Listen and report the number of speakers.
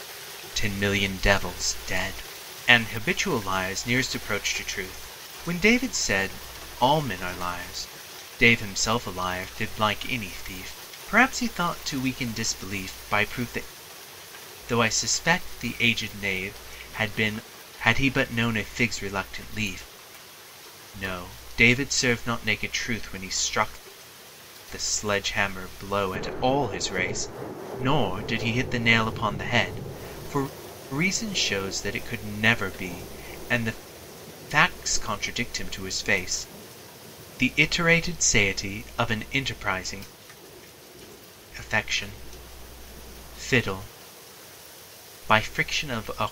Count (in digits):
1